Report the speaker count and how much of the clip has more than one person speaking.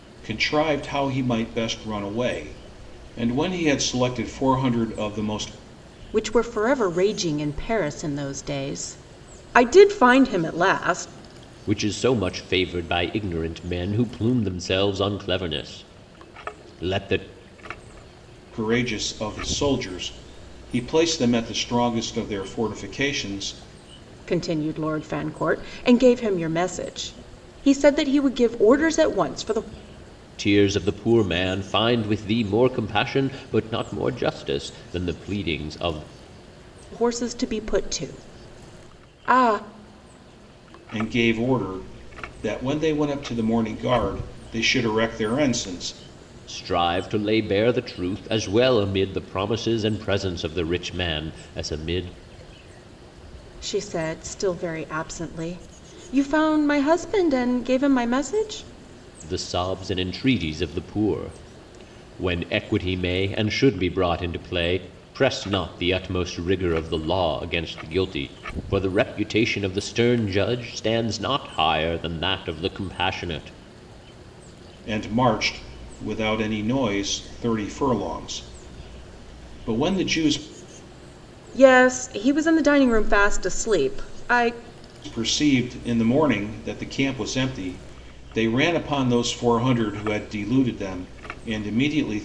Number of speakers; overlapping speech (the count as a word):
three, no overlap